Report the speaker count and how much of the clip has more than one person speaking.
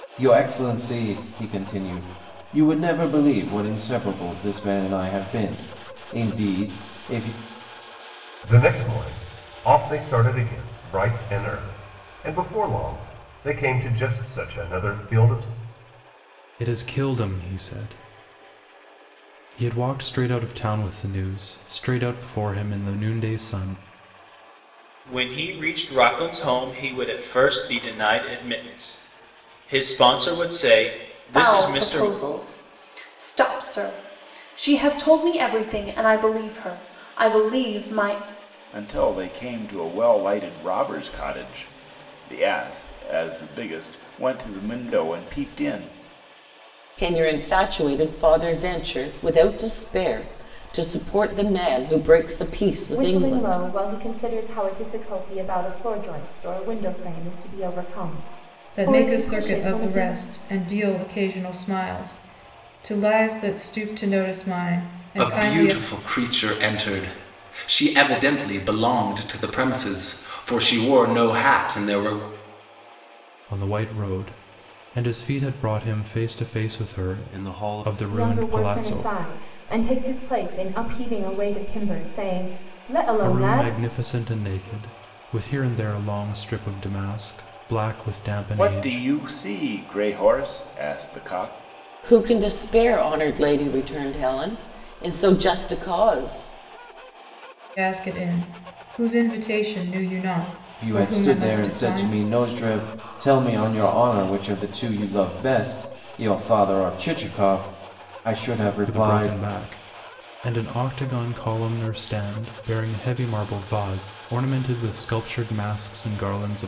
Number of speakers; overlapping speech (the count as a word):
ten, about 7%